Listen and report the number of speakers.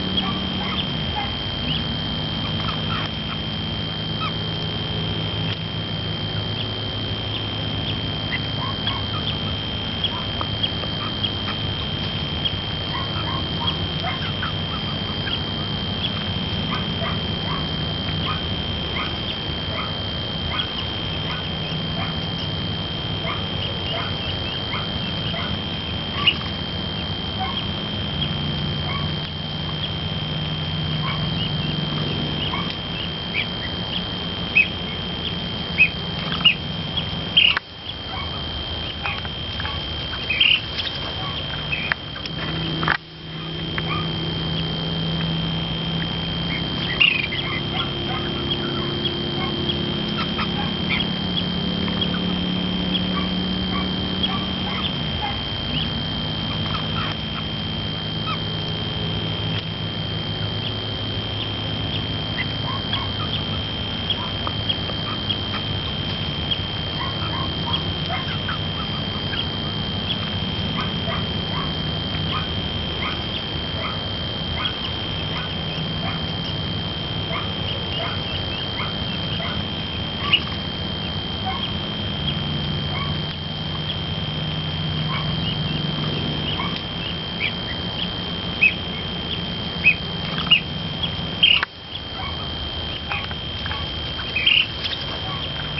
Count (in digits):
0